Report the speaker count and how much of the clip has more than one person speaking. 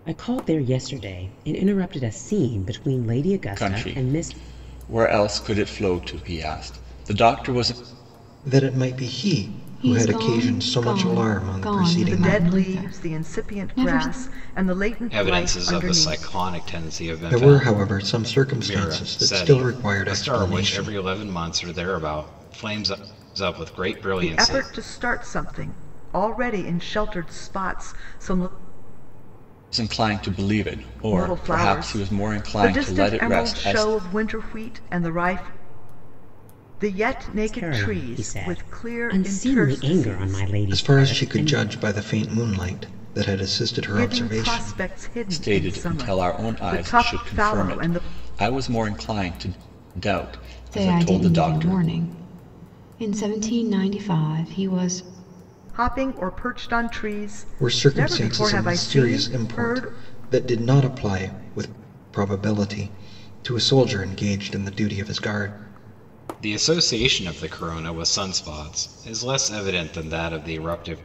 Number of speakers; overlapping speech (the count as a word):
six, about 34%